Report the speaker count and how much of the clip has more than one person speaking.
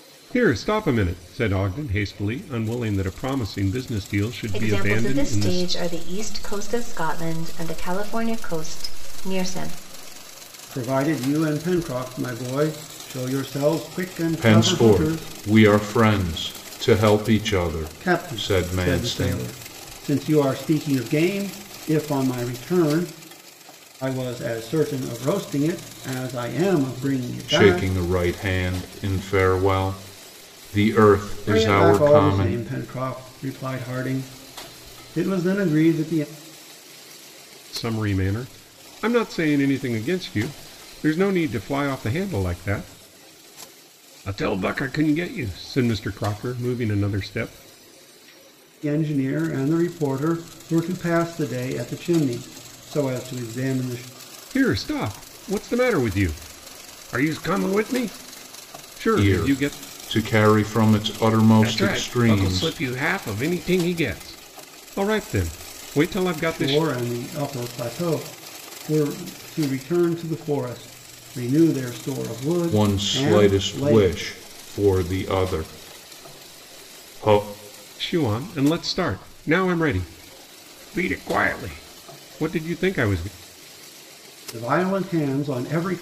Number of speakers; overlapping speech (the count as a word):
four, about 10%